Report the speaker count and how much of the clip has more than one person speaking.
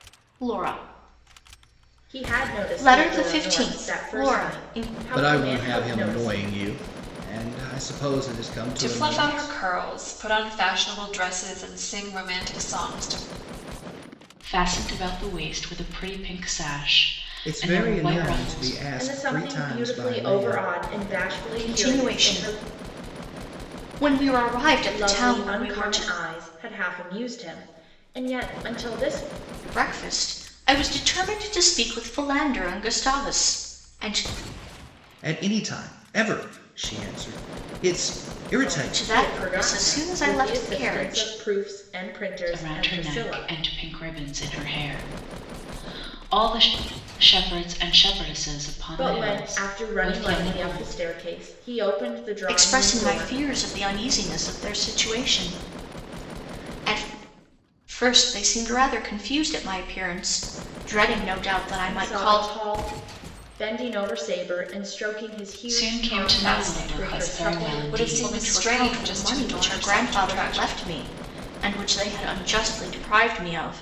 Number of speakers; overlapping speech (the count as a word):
five, about 31%